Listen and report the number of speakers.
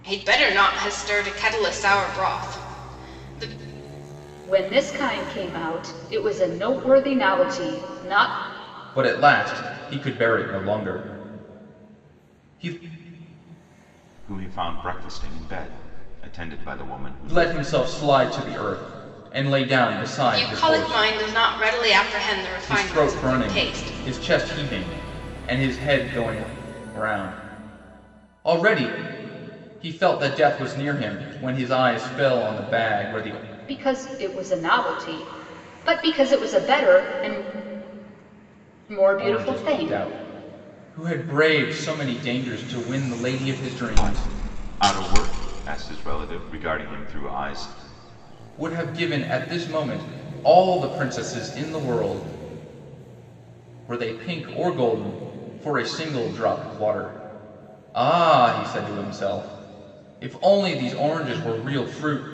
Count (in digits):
4